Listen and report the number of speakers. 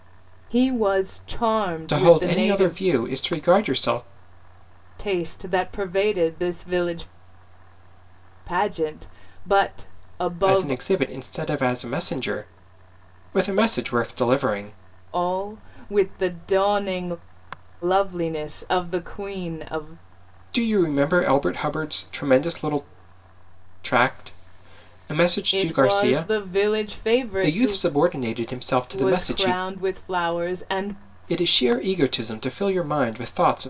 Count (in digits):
2